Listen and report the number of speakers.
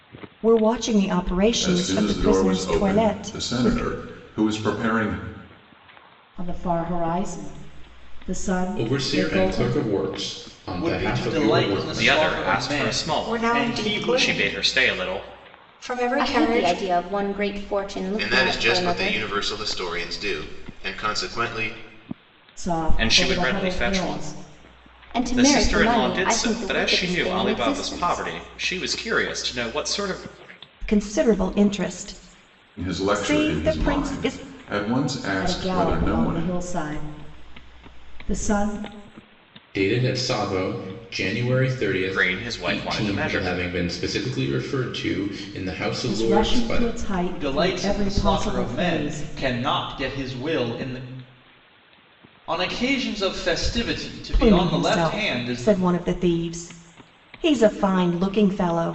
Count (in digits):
9